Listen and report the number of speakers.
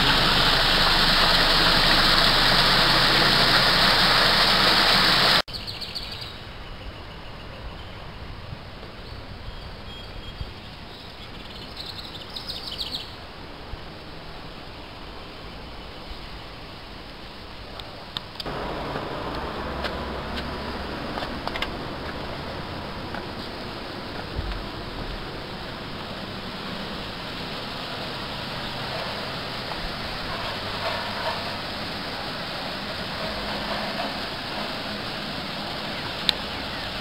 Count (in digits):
0